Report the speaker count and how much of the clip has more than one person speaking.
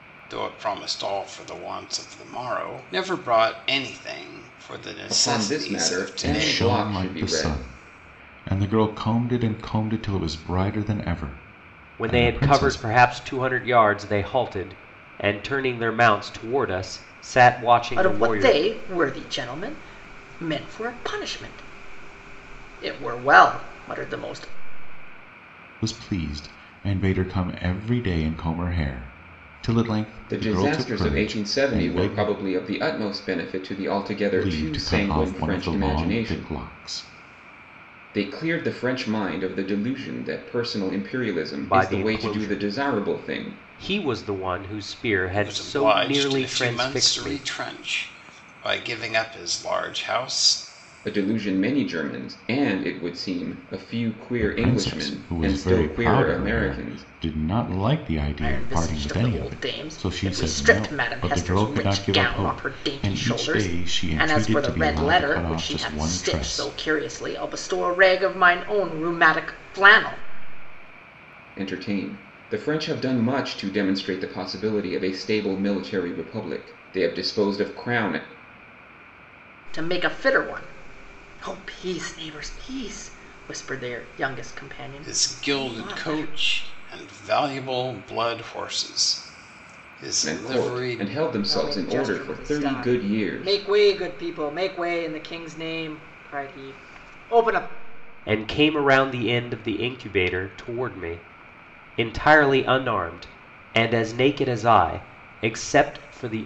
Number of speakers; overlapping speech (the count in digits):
5, about 26%